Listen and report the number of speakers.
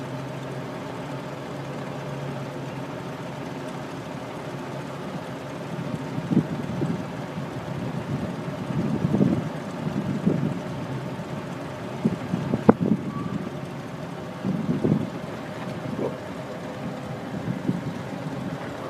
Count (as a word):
zero